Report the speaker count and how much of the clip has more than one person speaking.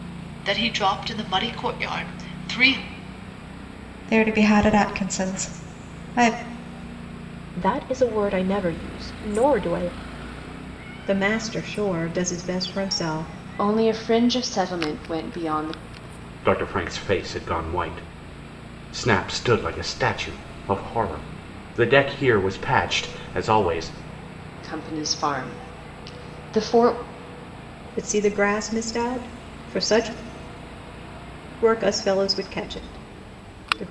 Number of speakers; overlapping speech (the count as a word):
six, no overlap